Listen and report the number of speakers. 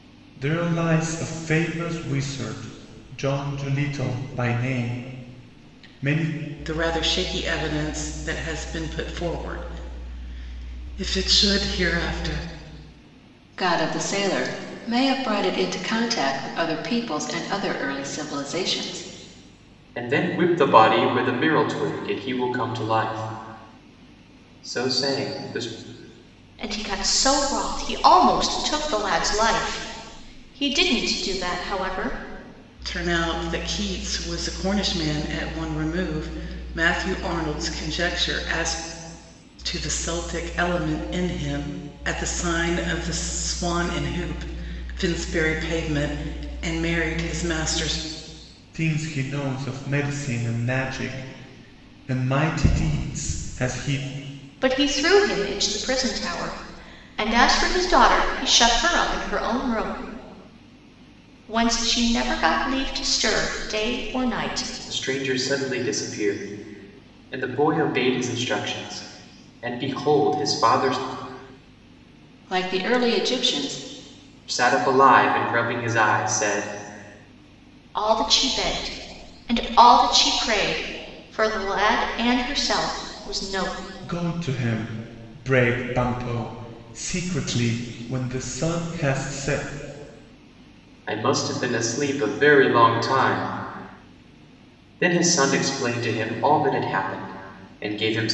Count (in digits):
5